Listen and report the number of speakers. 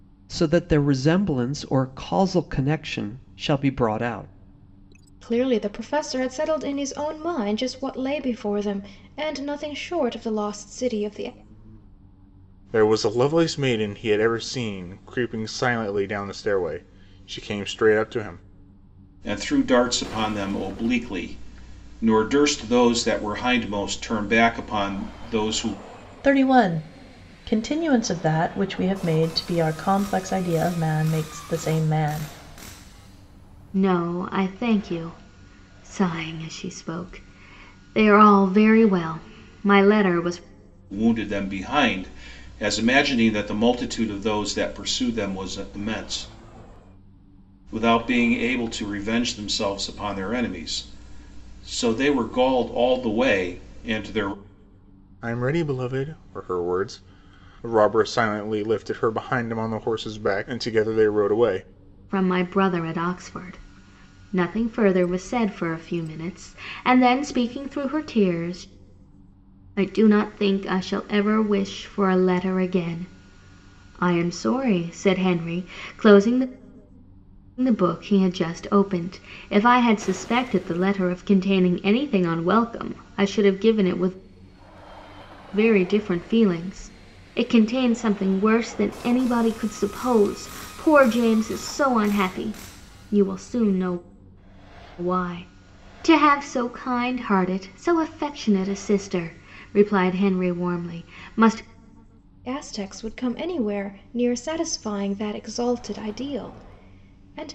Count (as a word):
six